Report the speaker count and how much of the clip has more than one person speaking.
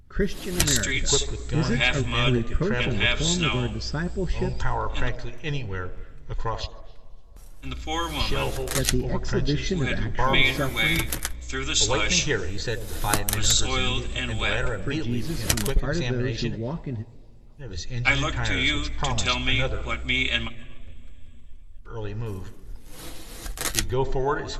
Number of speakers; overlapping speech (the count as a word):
three, about 54%